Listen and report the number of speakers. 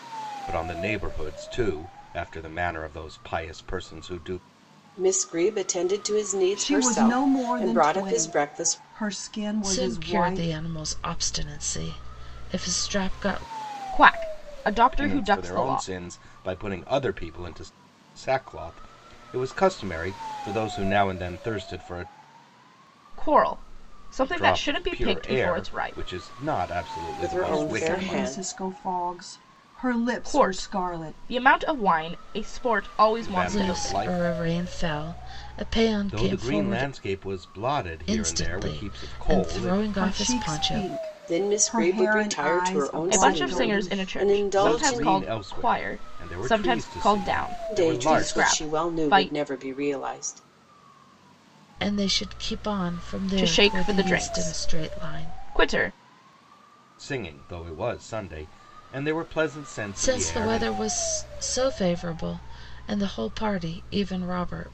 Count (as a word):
five